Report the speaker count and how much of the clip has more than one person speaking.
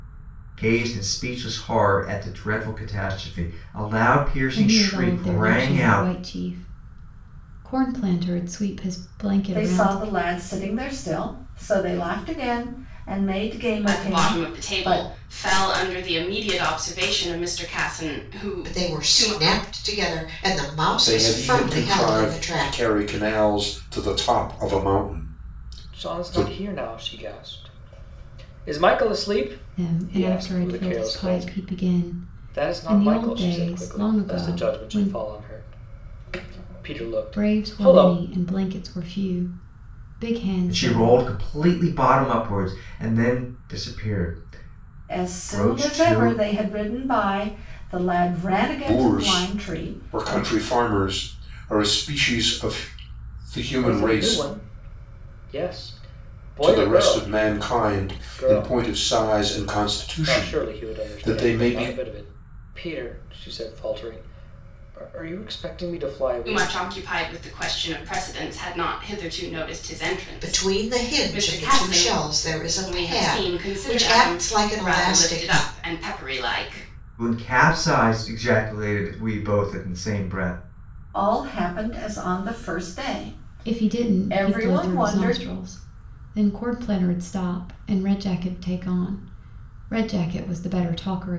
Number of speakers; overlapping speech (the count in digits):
7, about 31%